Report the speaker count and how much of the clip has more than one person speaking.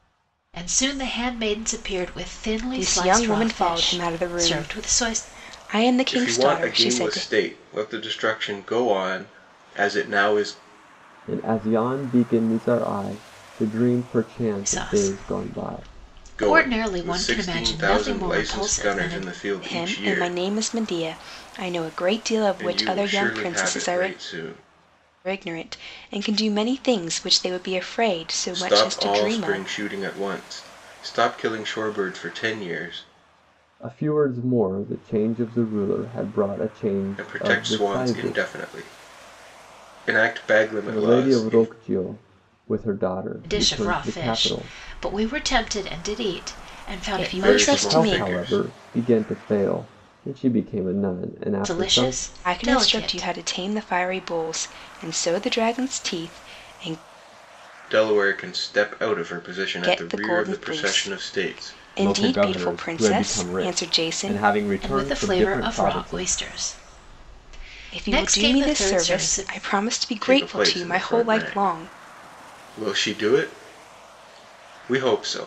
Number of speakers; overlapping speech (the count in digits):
4, about 36%